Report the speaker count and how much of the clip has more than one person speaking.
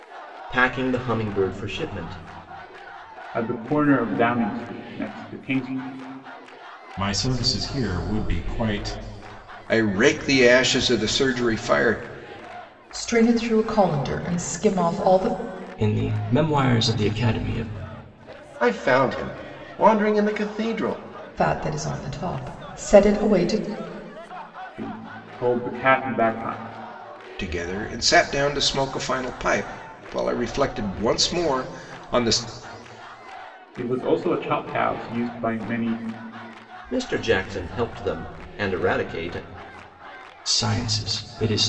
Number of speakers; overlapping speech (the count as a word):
seven, no overlap